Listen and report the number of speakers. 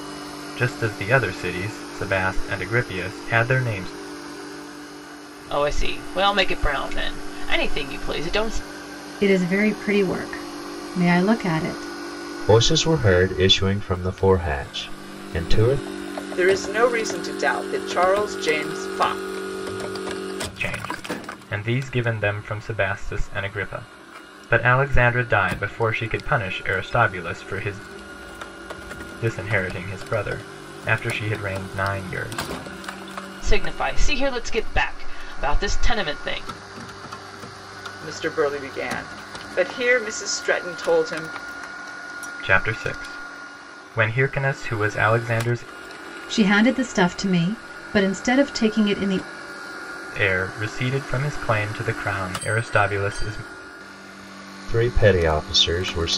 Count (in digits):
5